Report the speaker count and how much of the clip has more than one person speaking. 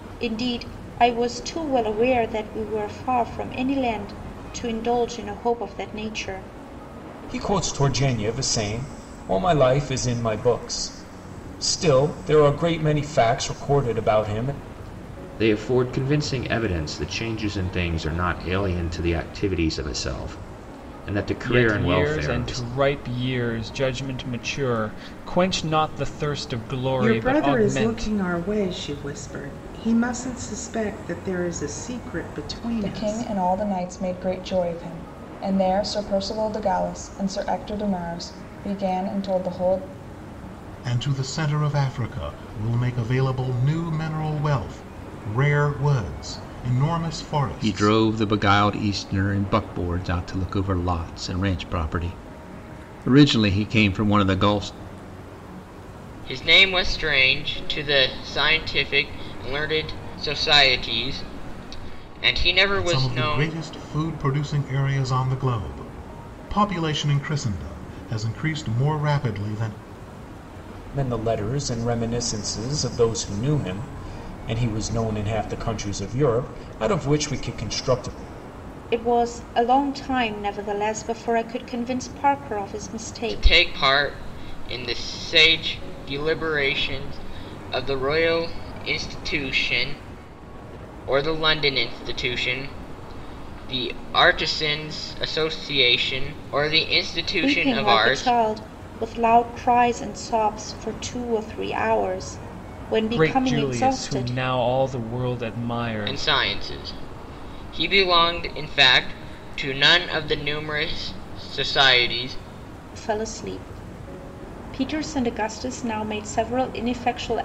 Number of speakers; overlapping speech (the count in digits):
9, about 6%